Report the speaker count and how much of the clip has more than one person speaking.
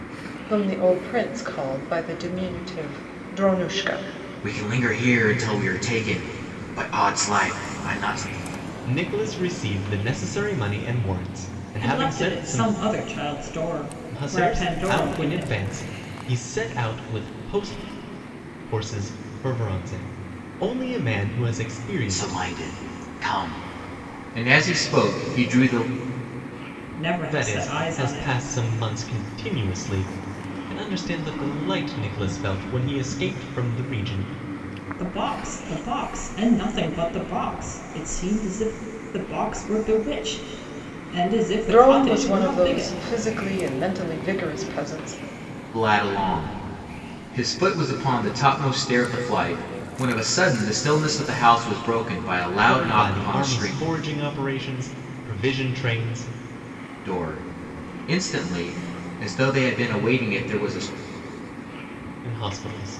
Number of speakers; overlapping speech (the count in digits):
4, about 10%